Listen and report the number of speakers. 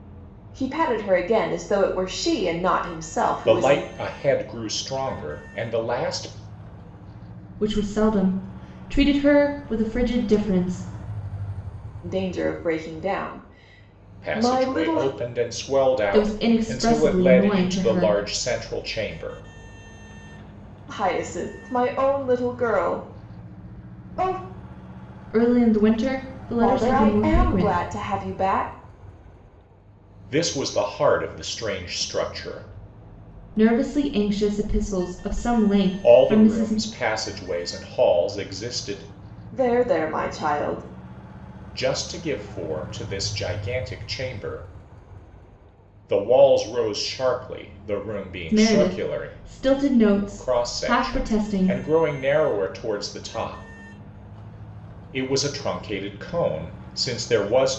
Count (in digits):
3